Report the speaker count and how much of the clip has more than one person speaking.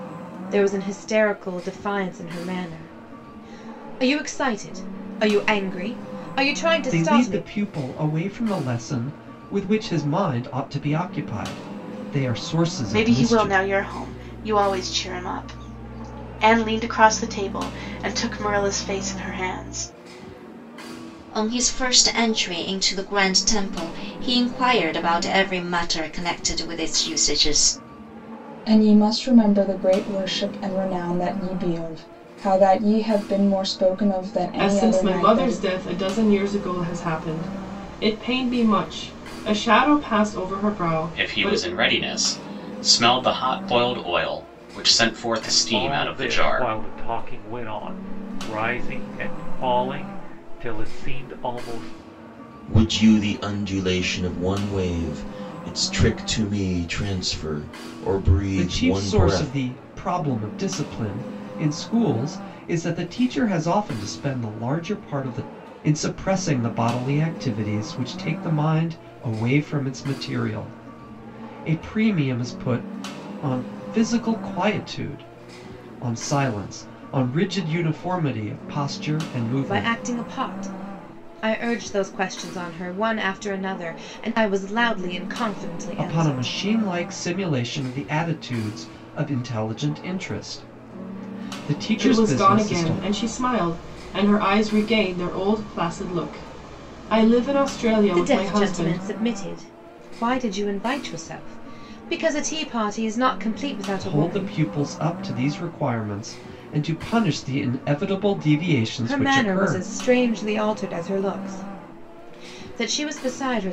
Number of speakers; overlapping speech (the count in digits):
9, about 9%